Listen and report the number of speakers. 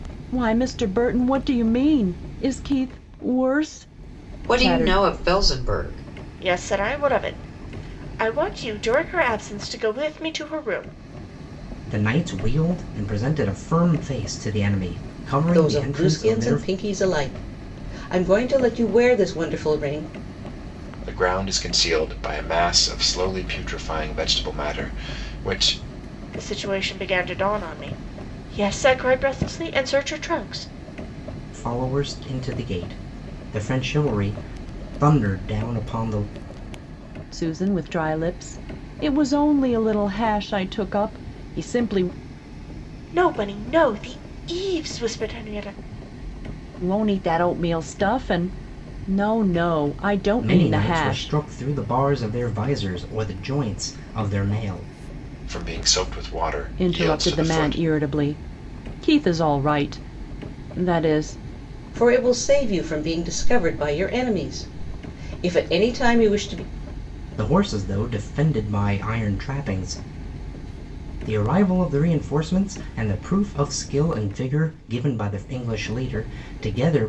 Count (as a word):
six